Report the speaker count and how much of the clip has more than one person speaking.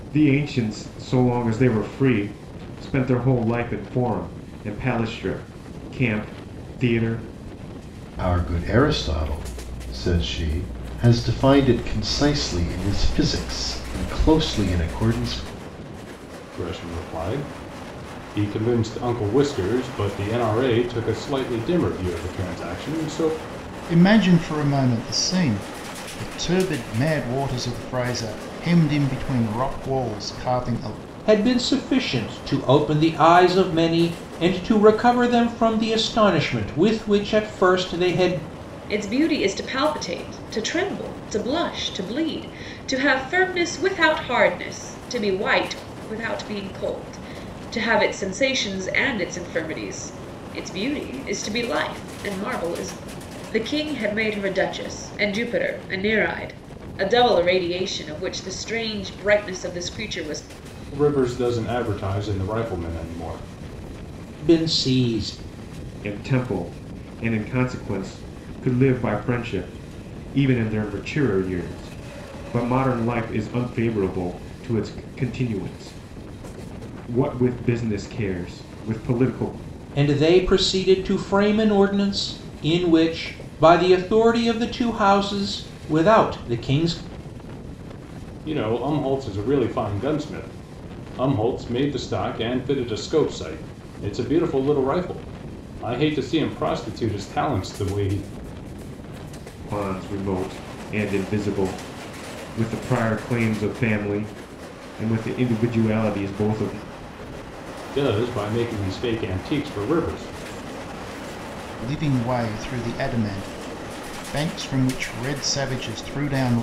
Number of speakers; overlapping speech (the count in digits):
6, no overlap